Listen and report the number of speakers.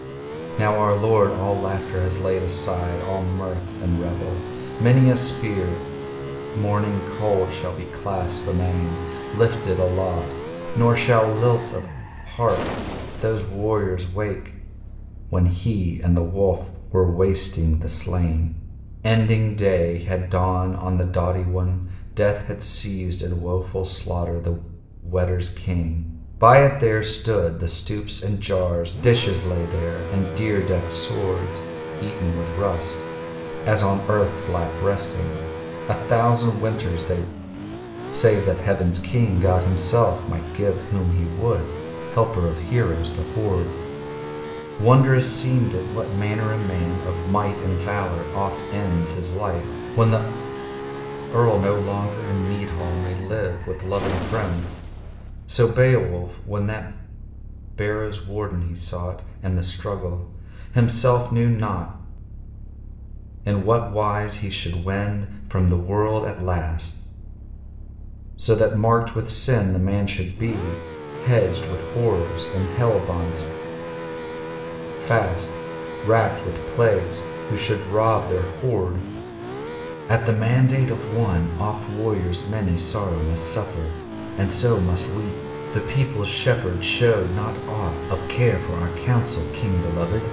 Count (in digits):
1